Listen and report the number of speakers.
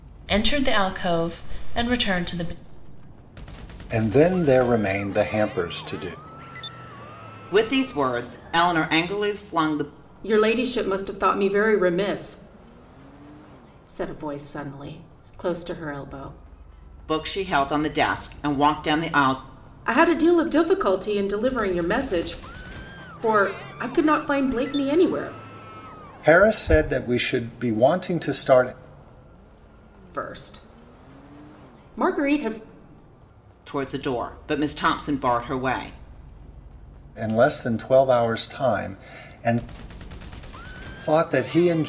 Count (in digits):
4